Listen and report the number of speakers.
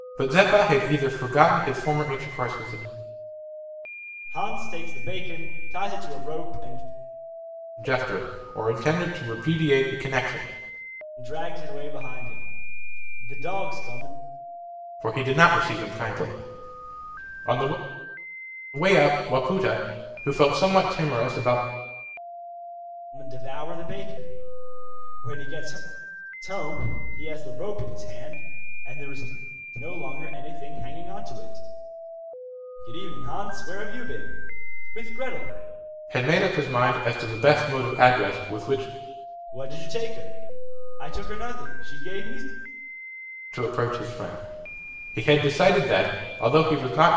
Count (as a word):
two